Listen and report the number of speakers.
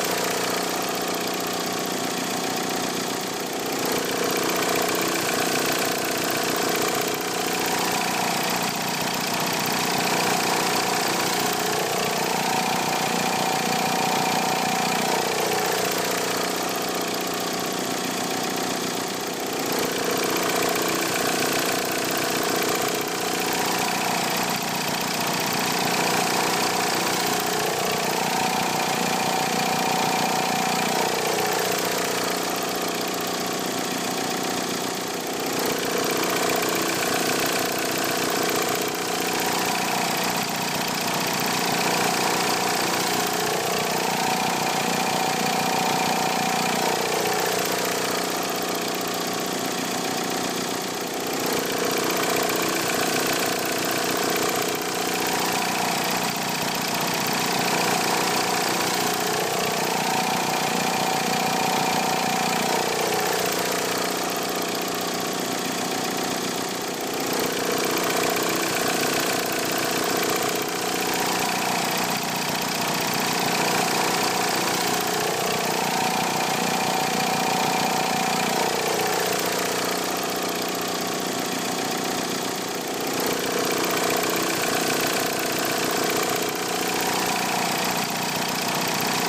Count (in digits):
0